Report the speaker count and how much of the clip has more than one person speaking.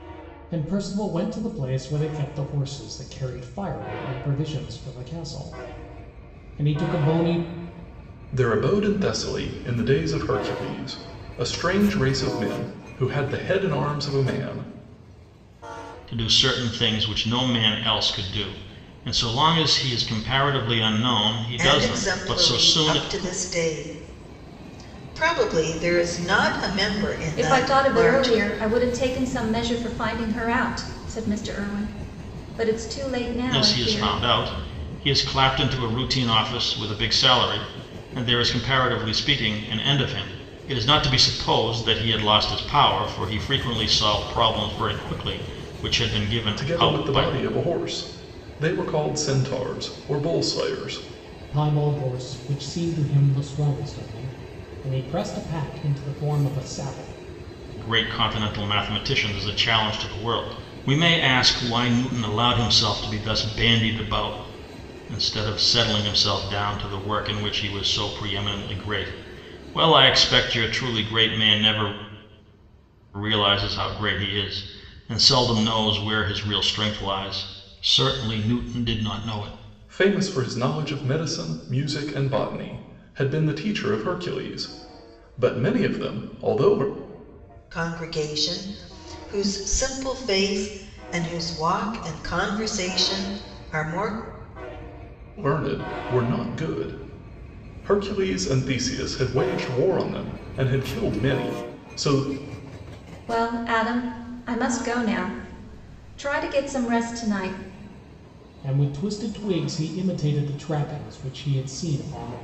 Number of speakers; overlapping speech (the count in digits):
5, about 4%